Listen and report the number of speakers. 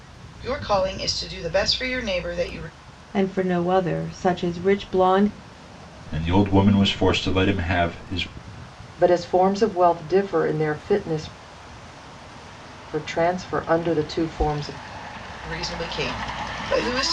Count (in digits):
4